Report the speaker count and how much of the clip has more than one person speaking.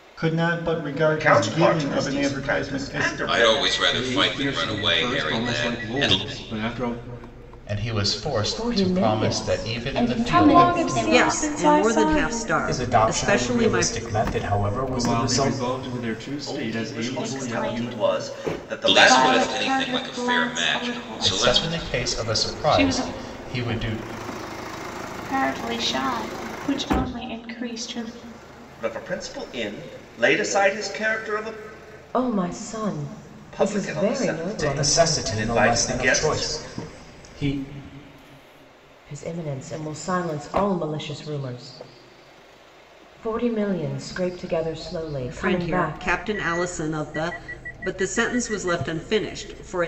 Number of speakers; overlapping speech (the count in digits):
10, about 43%